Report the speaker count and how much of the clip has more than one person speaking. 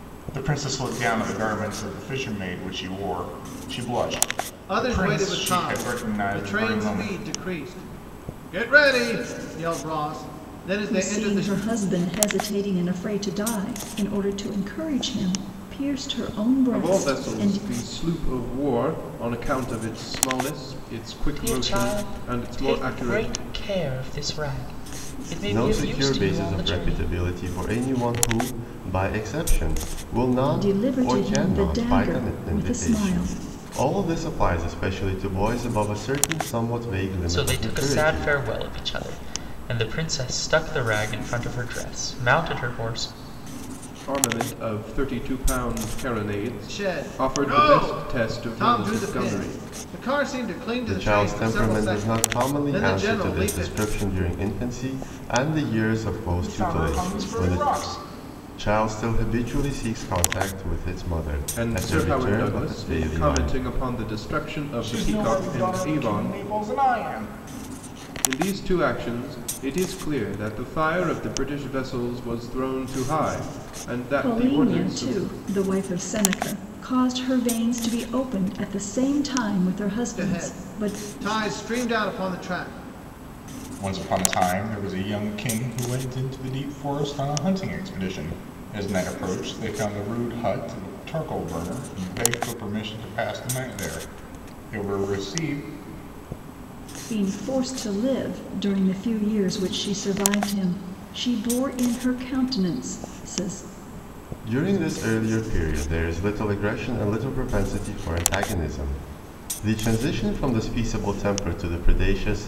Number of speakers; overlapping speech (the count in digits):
6, about 22%